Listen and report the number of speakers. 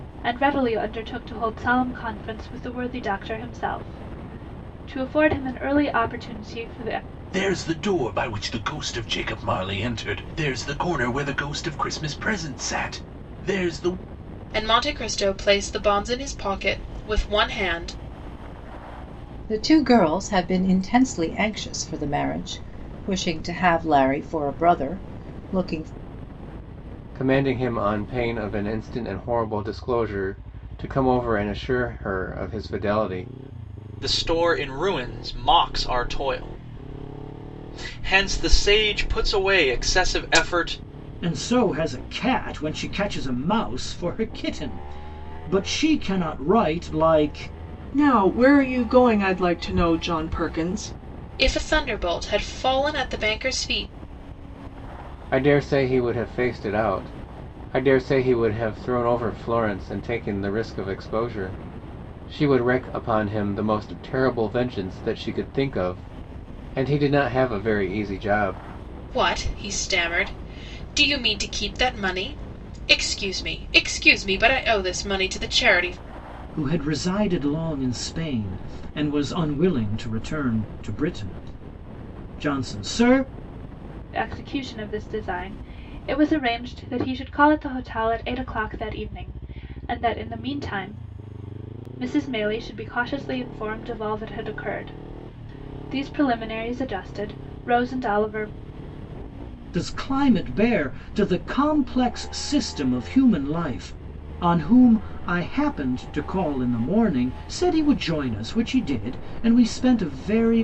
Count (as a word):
eight